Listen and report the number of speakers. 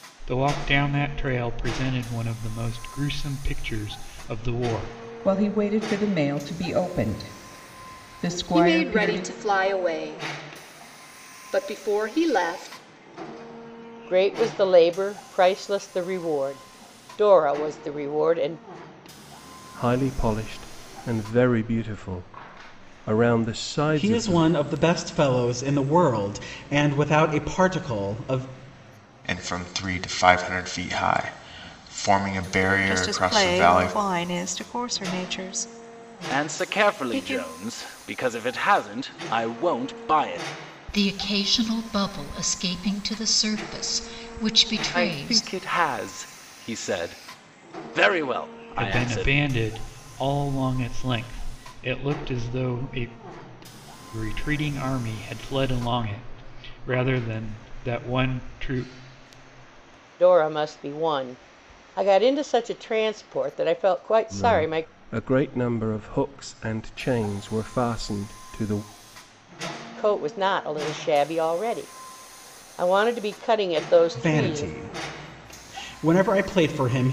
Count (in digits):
10